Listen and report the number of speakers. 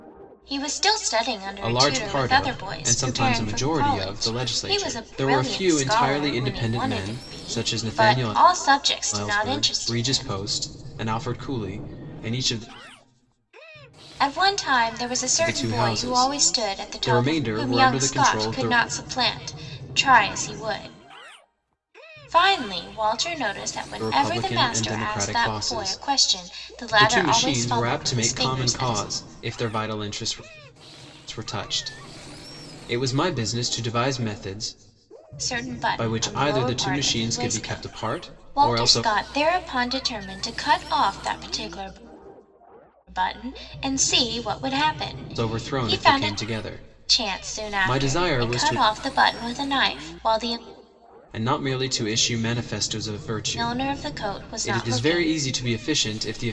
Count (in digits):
2